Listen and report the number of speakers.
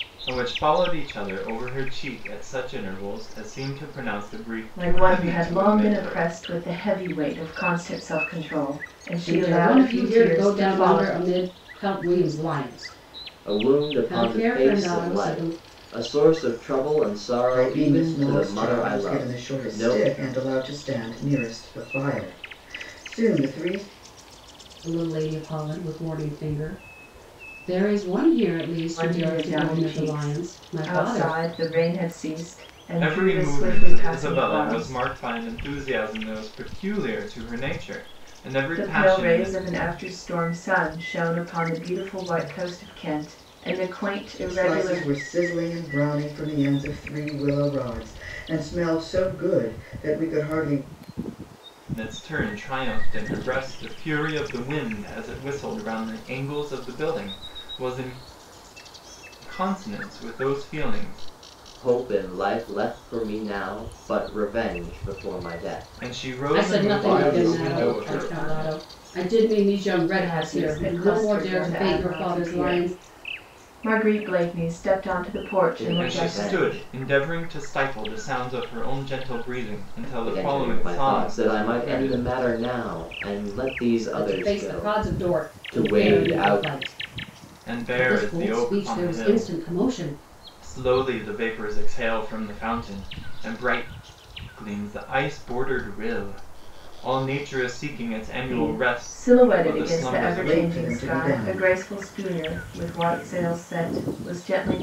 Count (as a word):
five